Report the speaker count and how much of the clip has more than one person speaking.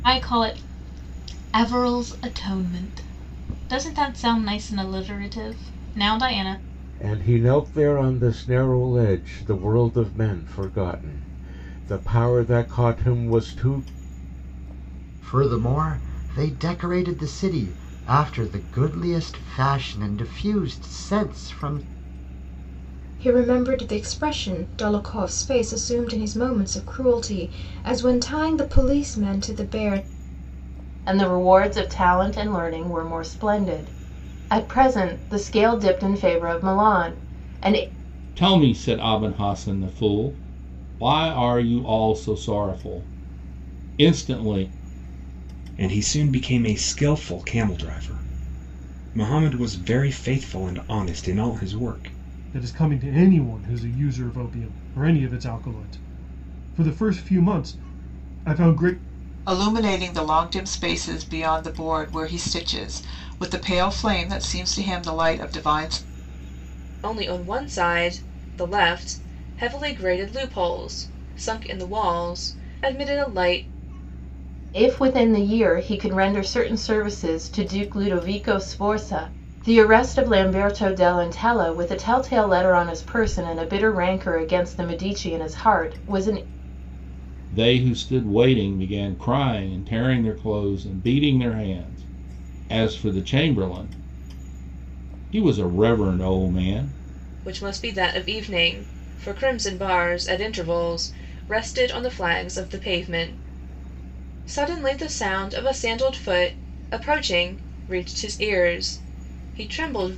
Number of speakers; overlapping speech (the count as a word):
ten, no overlap